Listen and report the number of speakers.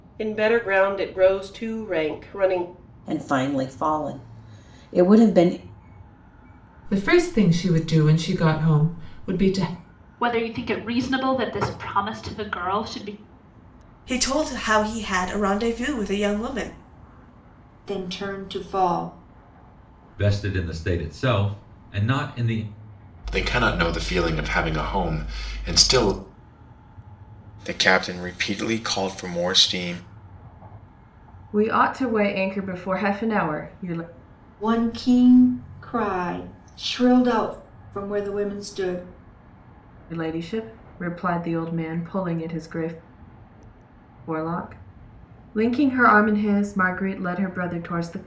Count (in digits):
10